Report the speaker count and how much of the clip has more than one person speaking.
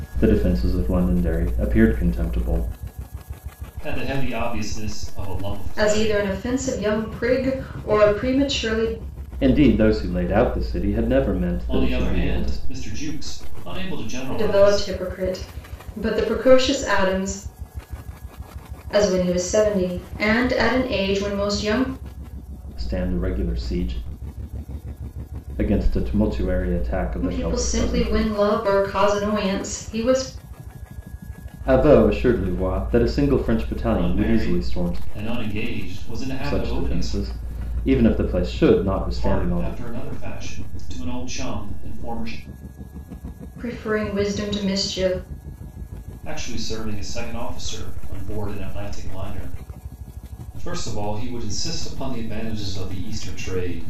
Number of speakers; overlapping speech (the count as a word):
three, about 10%